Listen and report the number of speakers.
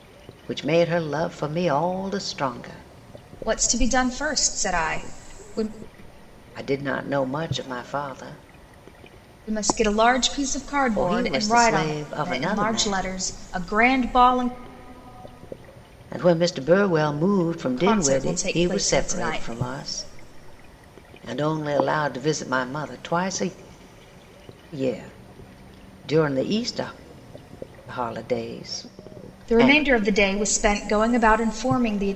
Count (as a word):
two